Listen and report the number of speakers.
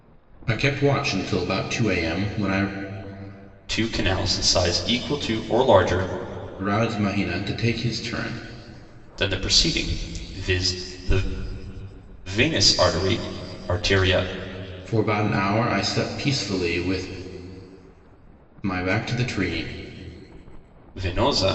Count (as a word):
two